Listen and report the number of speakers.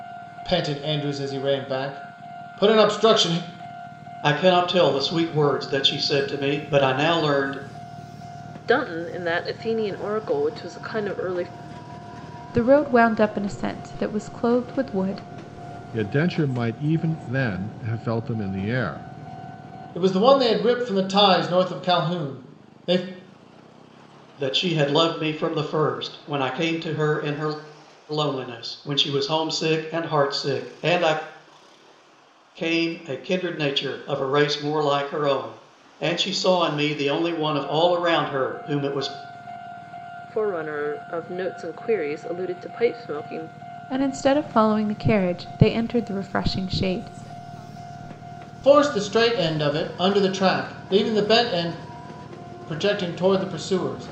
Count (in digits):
5